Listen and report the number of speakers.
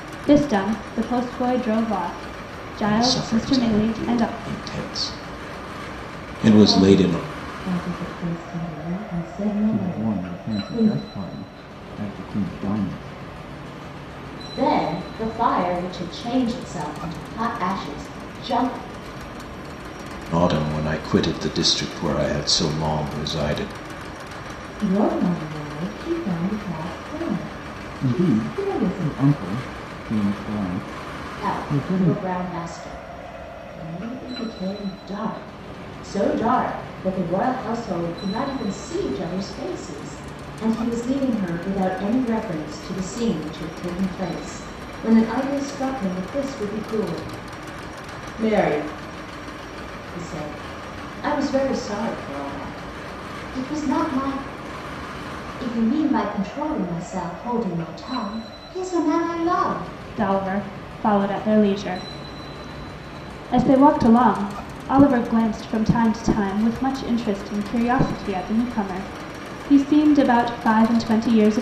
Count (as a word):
five